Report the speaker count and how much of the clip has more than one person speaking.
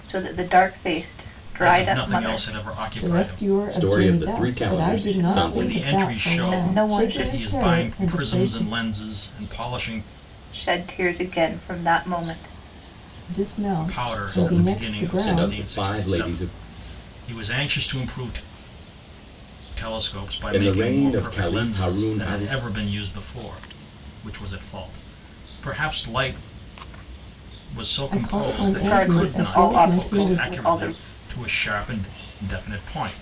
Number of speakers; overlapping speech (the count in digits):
4, about 42%